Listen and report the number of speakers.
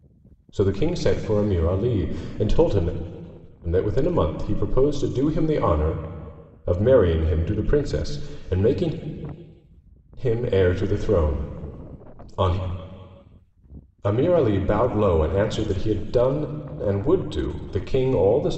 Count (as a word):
one